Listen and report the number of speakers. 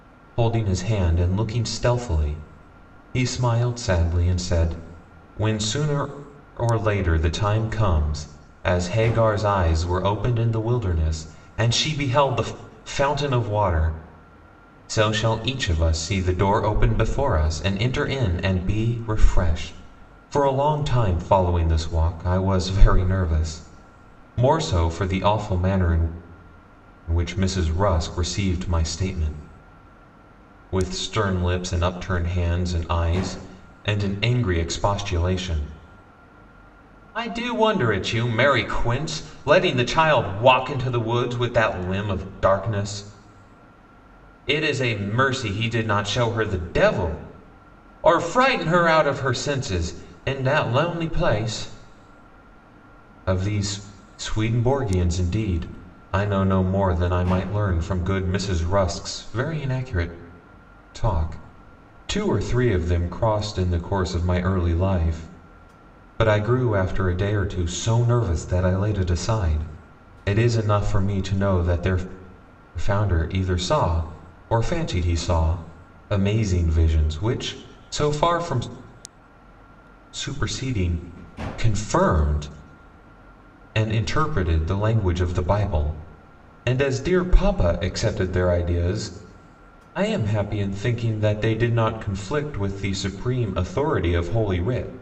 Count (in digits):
1